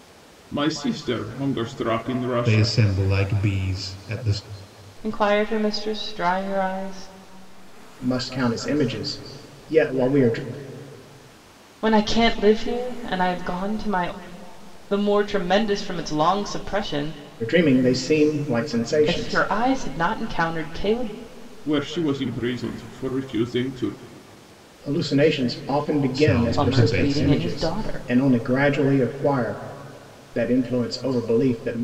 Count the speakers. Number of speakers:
4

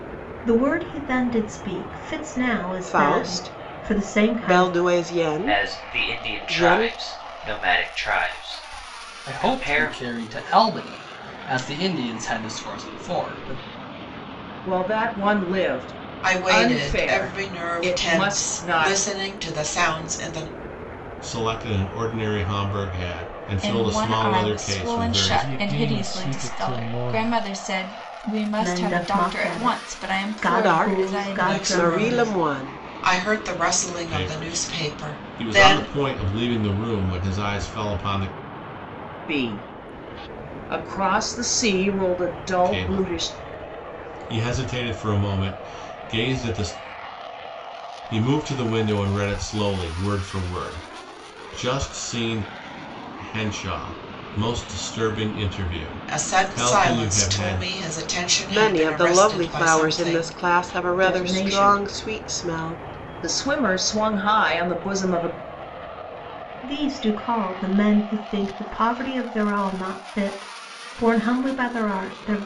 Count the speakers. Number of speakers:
9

